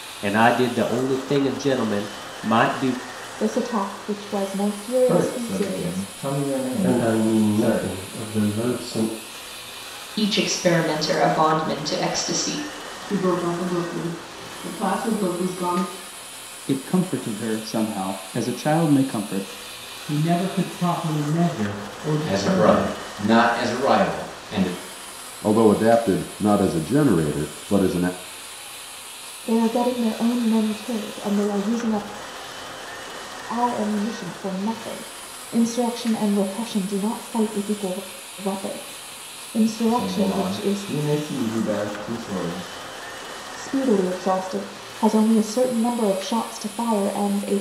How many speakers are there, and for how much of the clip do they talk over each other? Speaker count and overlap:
ten, about 8%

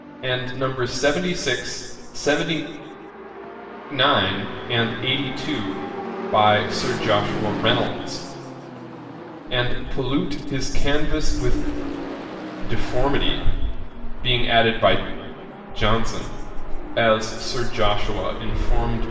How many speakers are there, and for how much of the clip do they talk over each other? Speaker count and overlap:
one, no overlap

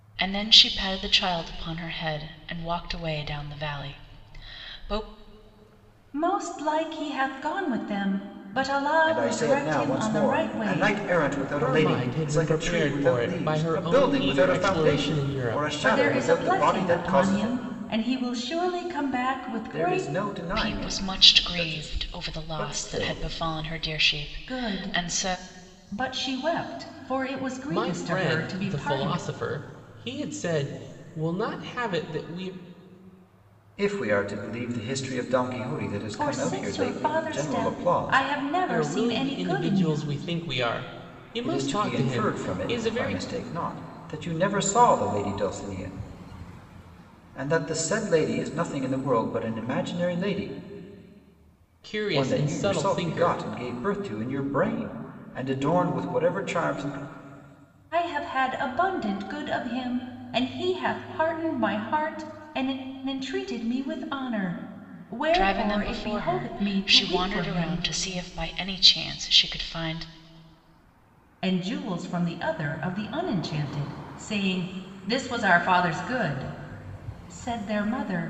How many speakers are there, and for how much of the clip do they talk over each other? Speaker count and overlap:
four, about 30%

